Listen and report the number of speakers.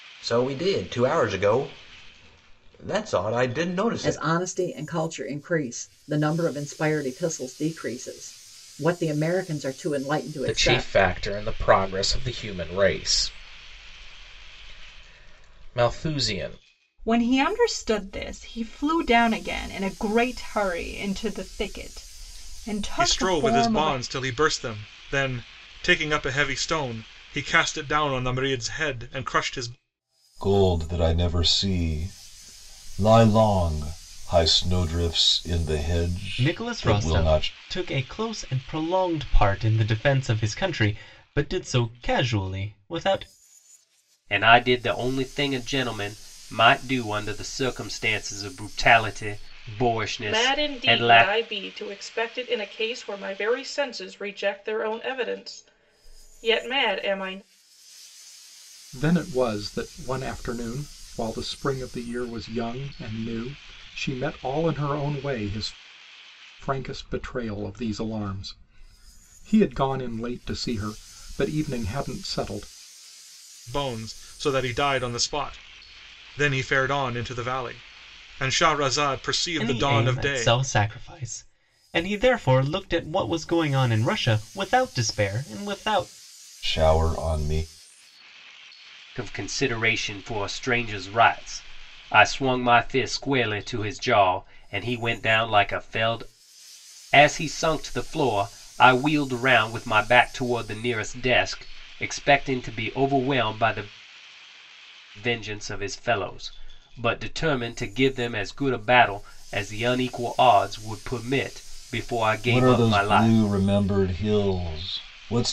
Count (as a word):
ten